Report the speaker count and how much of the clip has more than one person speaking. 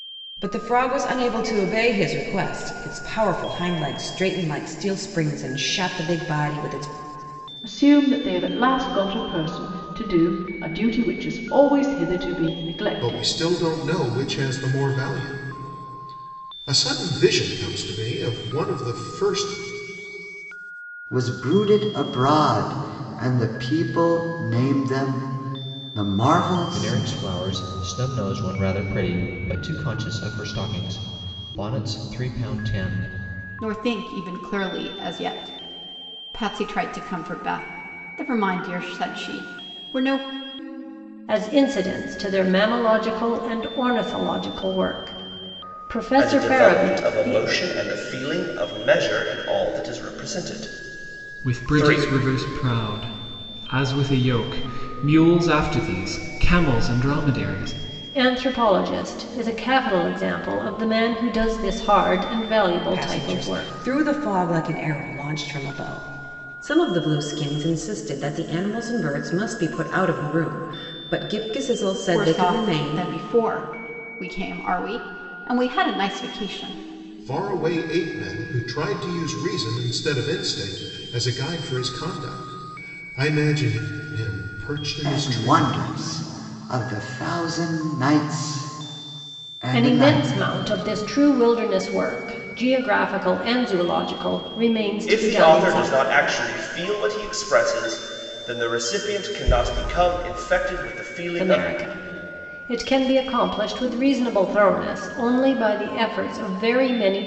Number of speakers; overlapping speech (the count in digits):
9, about 7%